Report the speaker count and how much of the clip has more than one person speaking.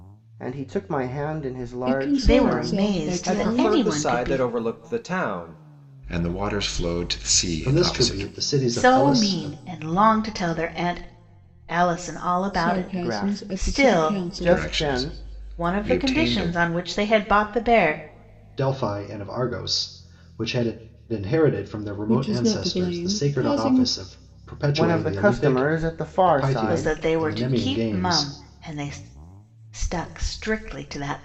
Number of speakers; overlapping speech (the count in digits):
6, about 41%